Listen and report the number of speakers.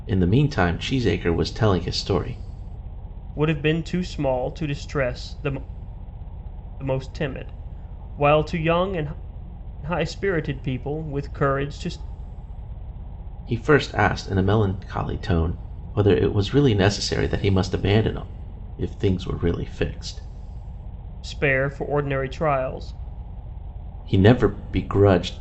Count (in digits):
2